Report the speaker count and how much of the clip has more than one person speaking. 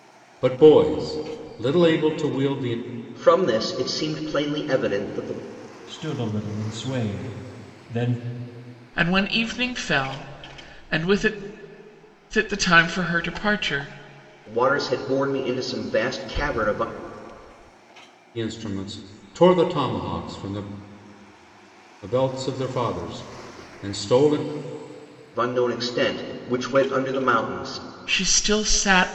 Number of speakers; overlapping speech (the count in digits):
4, no overlap